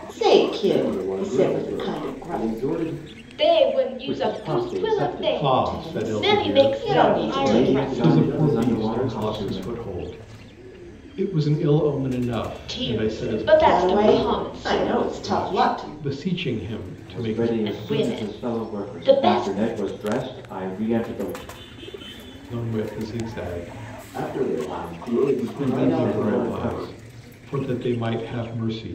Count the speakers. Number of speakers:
5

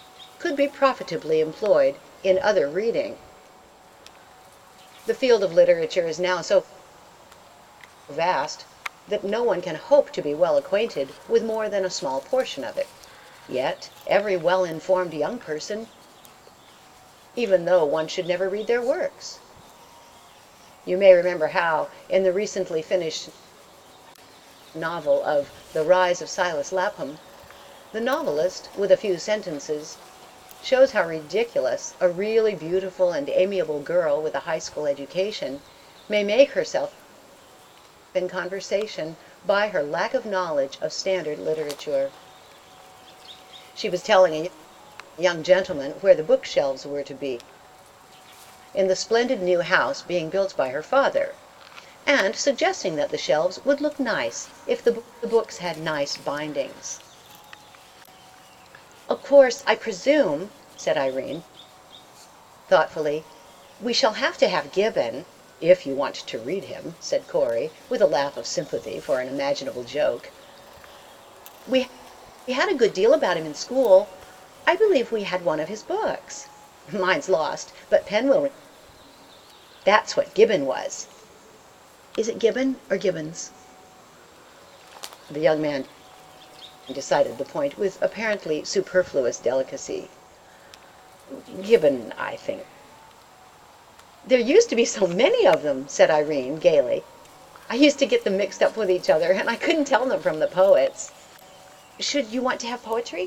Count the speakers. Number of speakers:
1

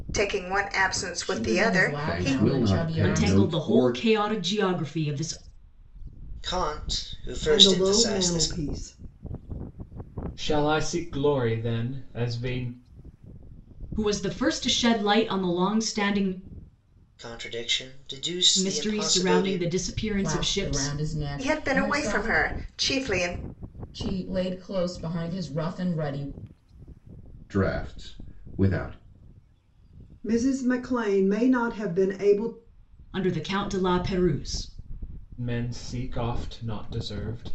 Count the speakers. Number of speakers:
7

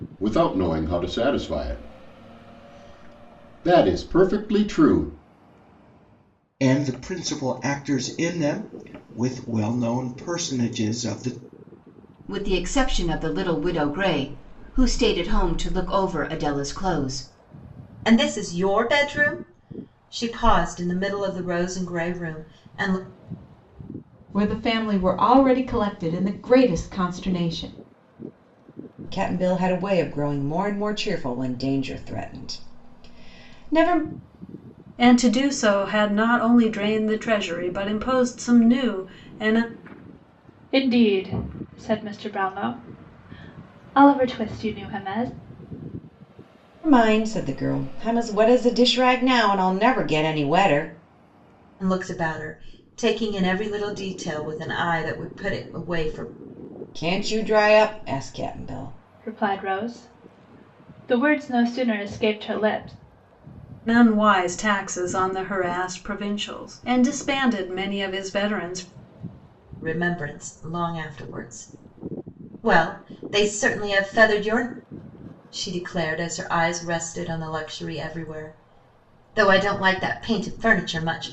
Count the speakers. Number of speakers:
8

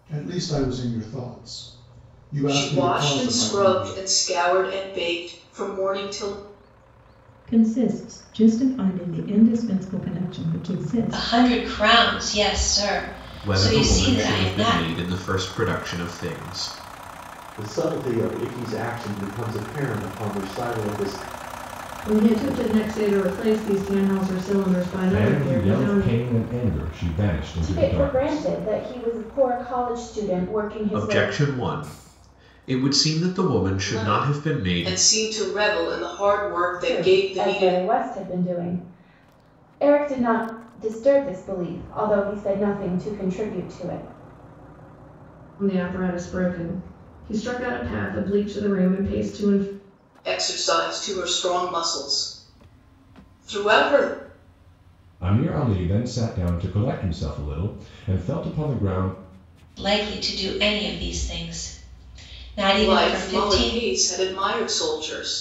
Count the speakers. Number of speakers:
9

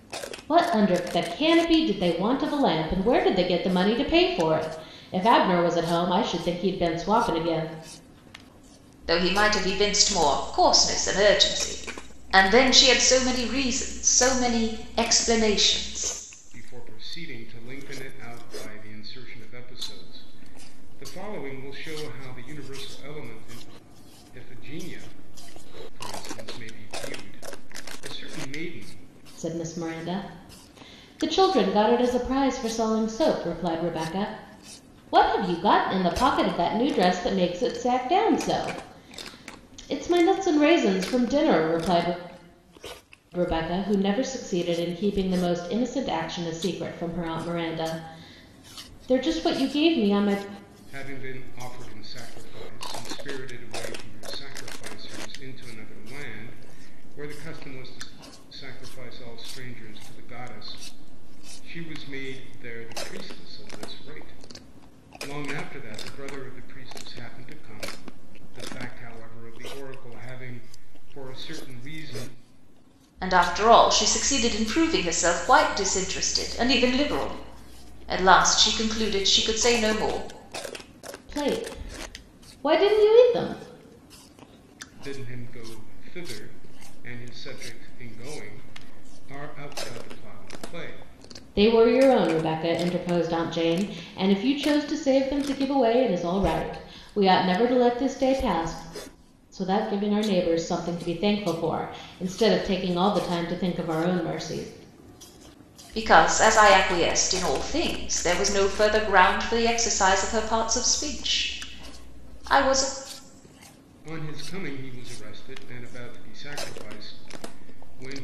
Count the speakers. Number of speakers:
3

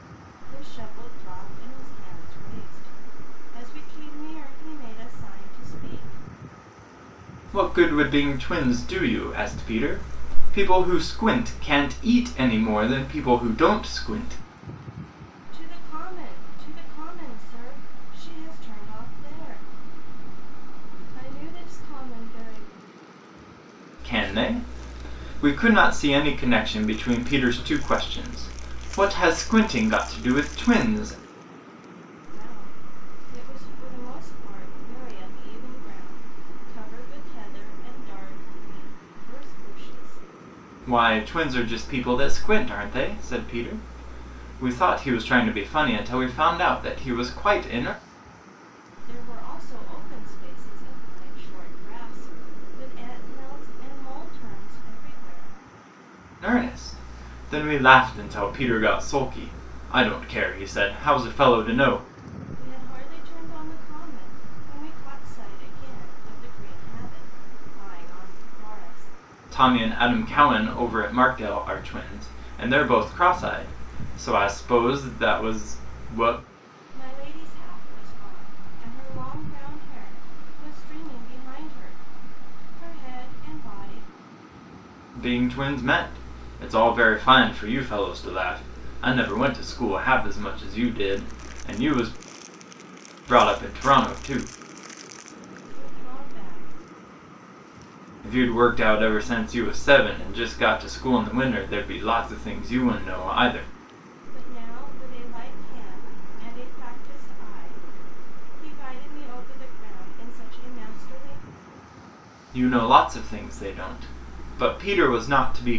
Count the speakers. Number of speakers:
2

